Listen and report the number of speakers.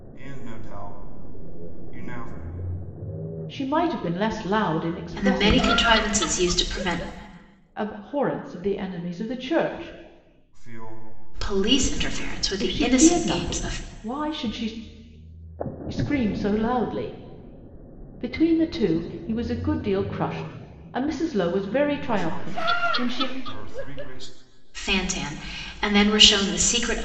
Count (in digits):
3